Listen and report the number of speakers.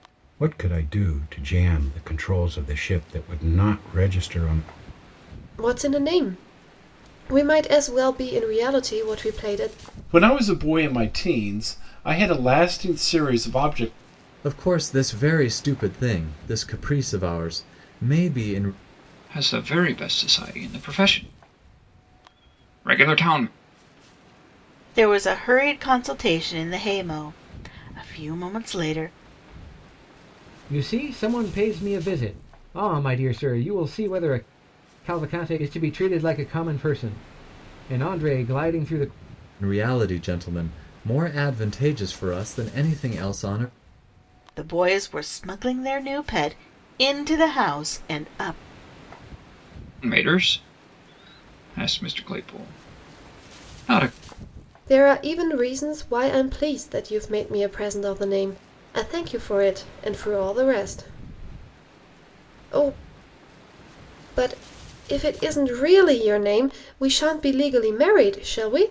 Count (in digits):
7